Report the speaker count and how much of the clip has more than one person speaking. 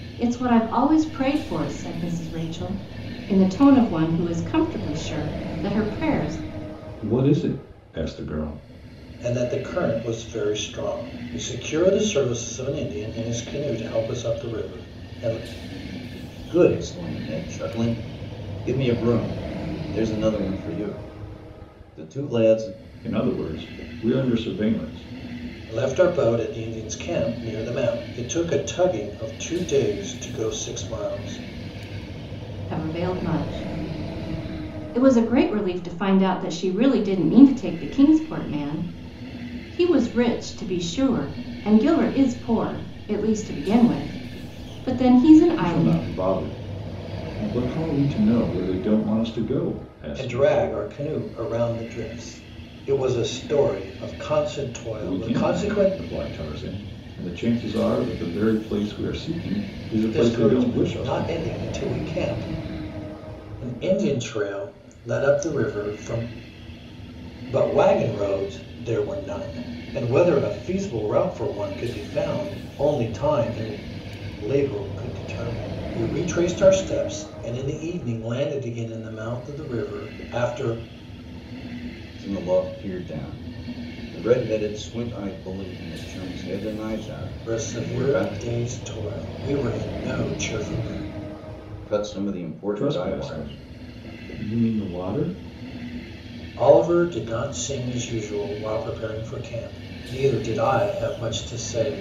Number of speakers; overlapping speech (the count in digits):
4, about 5%